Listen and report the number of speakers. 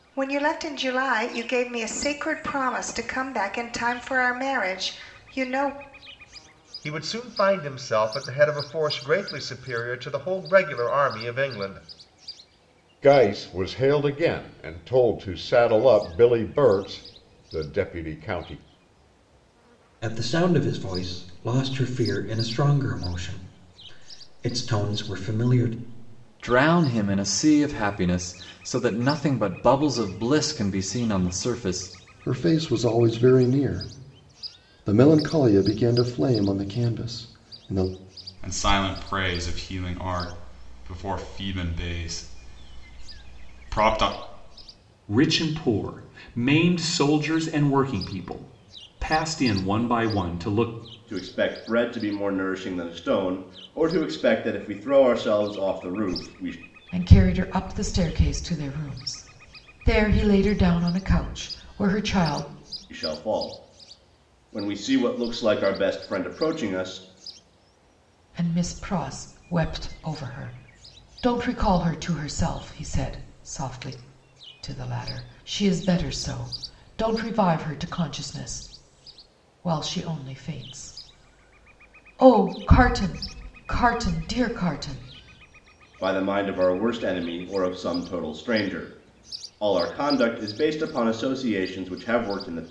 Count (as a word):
ten